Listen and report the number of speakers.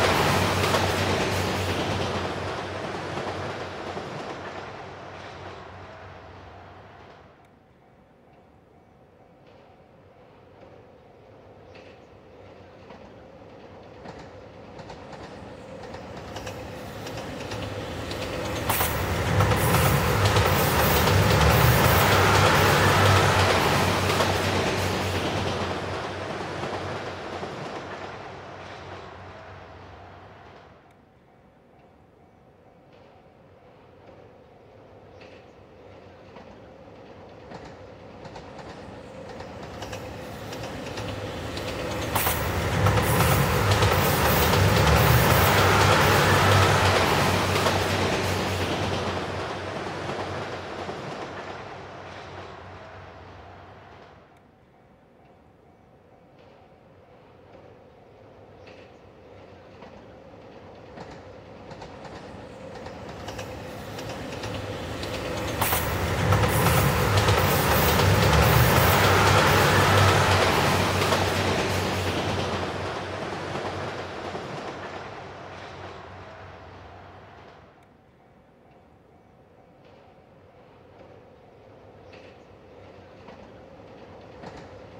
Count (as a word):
zero